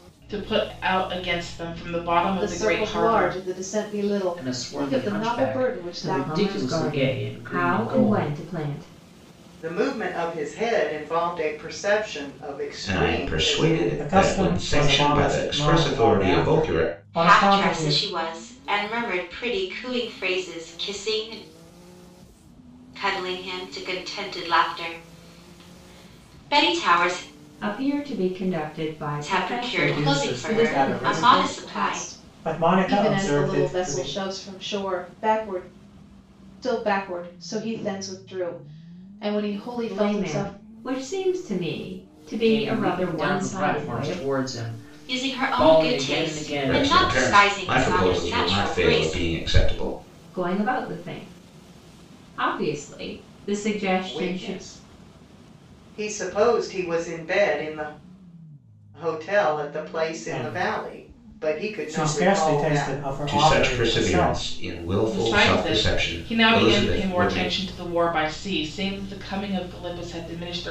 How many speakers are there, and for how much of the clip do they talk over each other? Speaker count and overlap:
eight, about 41%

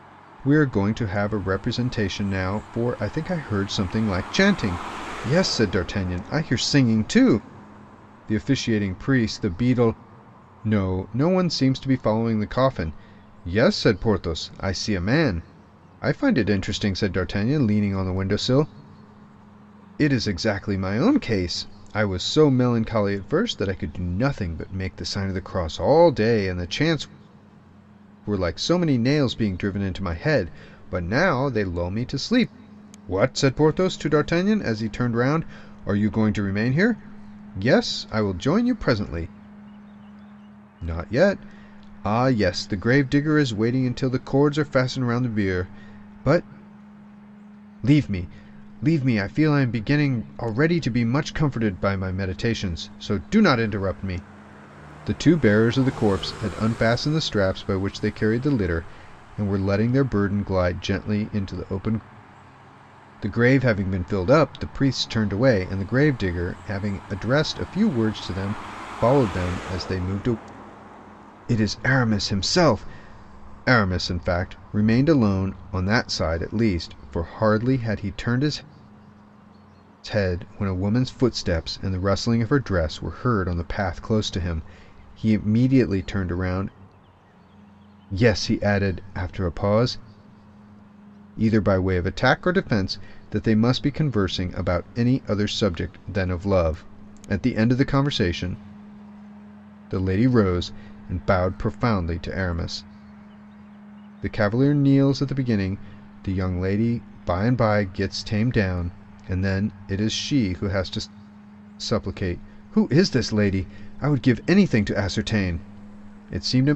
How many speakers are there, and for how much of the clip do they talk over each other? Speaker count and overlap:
one, no overlap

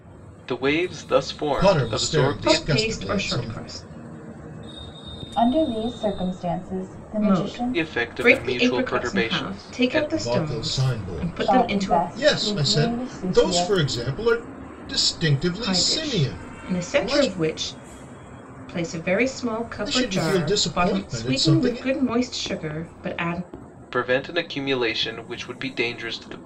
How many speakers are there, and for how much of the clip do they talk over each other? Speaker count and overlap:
four, about 47%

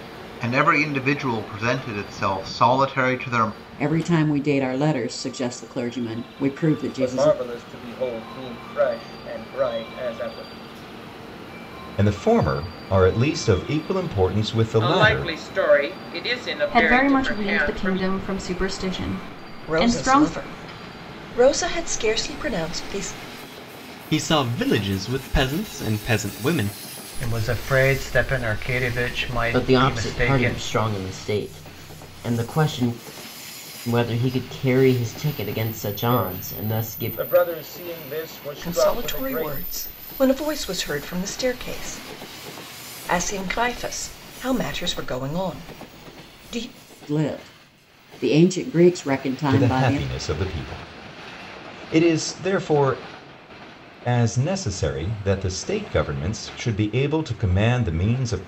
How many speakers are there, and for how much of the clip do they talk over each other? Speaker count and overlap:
ten, about 12%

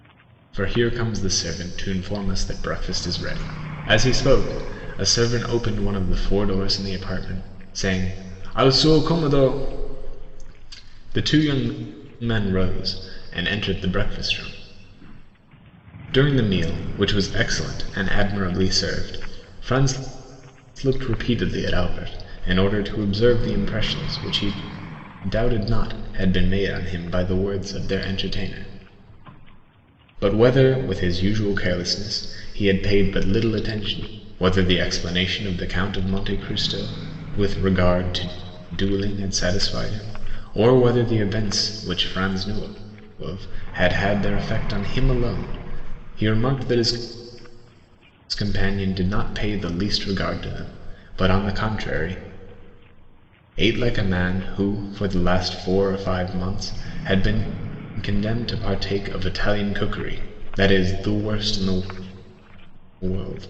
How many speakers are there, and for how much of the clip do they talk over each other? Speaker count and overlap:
one, no overlap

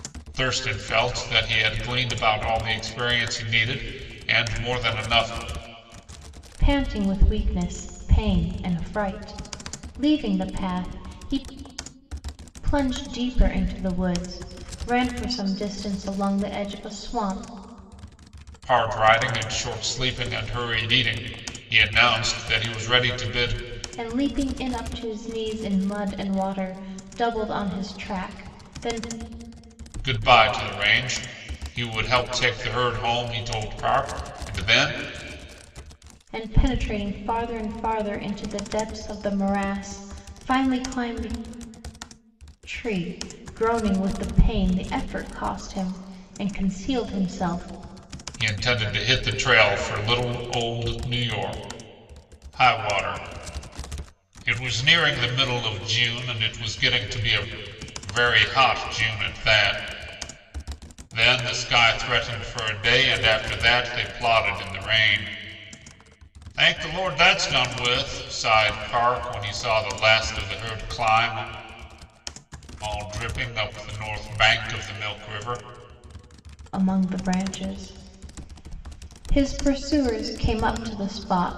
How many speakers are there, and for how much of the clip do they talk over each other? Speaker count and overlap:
two, no overlap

